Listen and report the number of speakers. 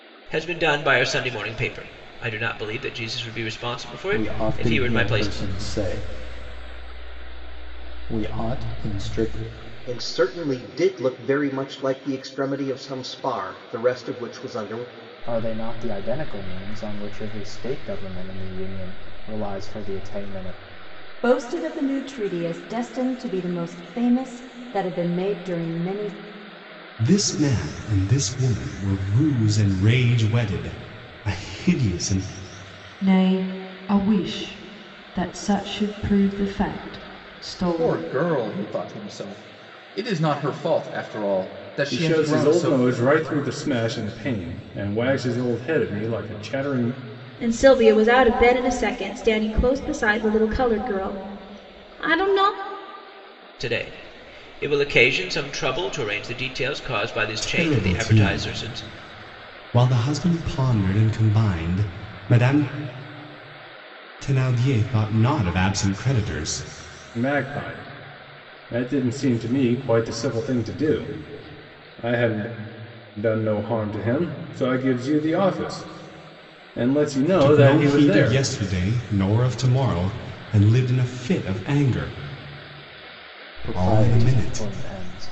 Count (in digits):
10